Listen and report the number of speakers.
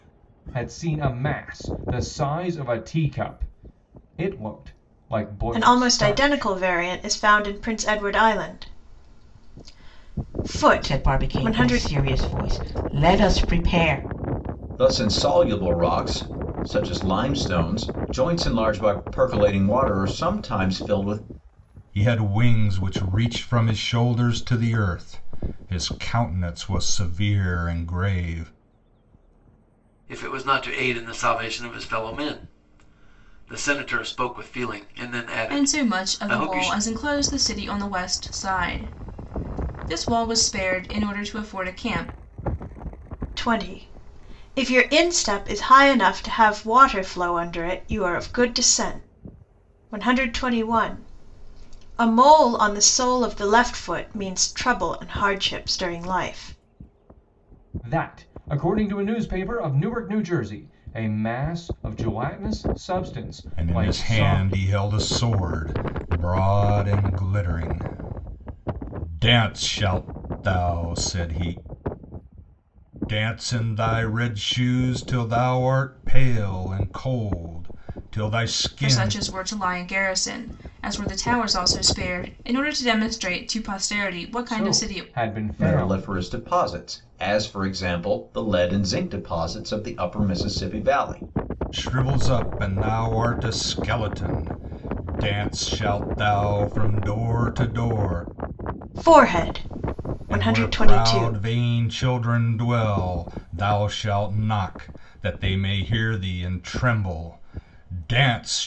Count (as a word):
seven